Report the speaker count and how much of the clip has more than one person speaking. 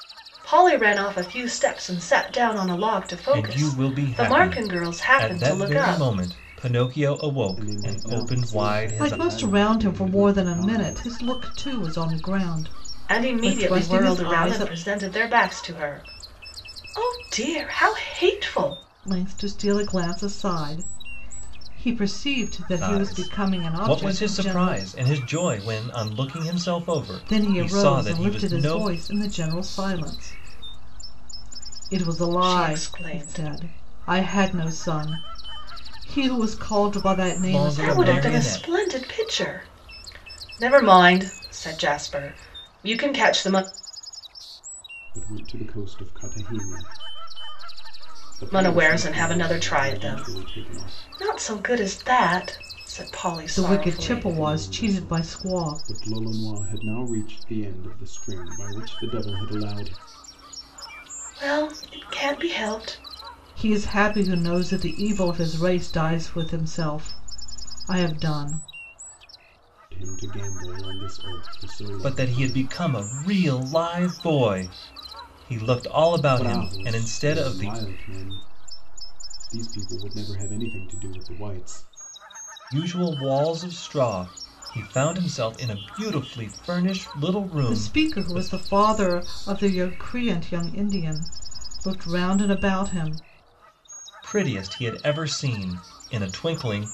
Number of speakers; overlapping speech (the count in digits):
4, about 23%